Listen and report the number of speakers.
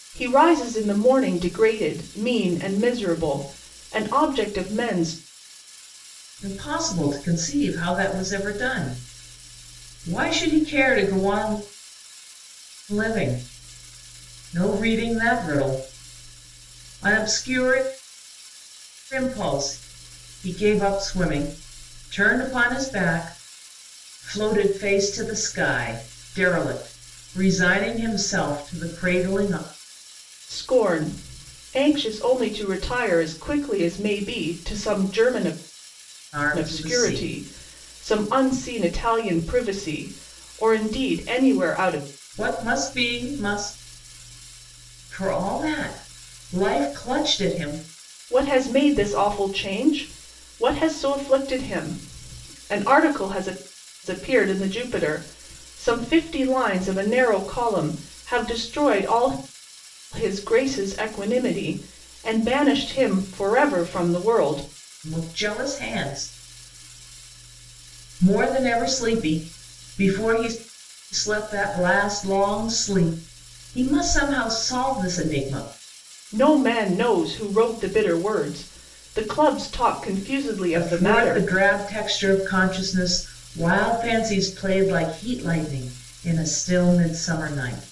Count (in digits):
2